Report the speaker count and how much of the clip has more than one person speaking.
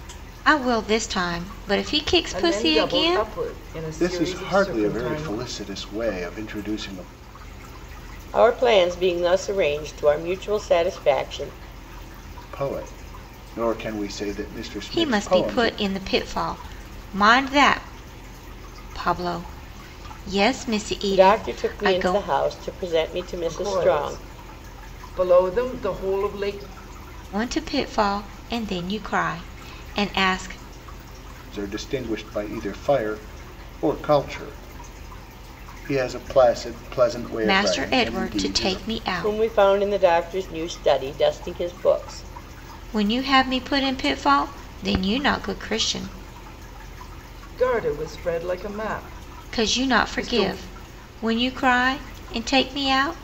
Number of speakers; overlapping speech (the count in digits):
4, about 15%